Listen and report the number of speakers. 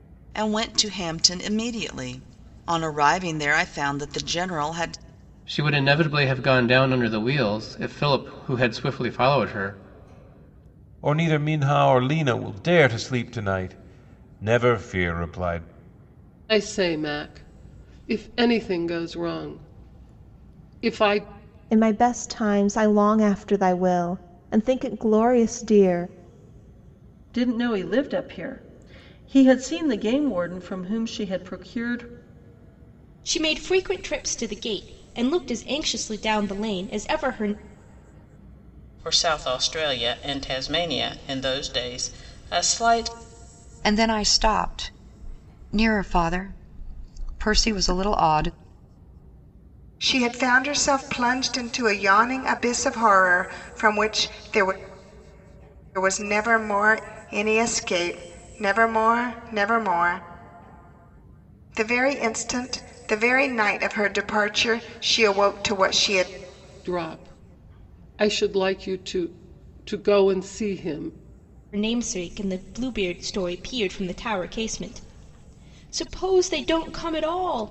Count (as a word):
ten